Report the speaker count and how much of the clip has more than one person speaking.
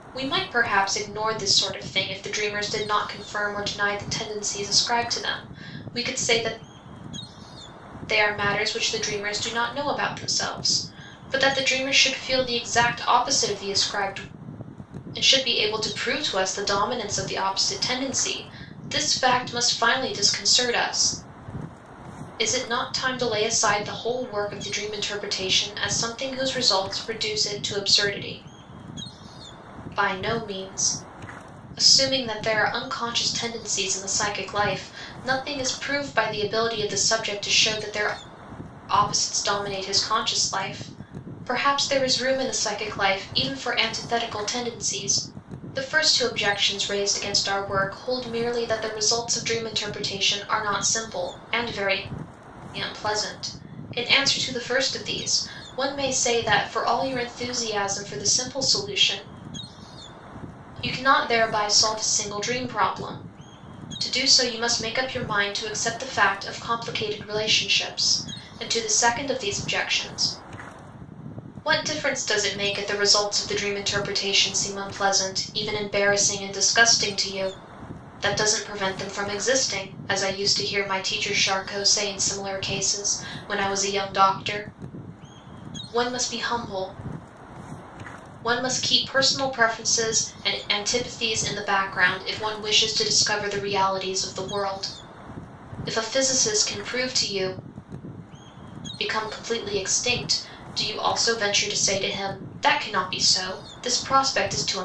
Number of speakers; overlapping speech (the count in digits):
1, no overlap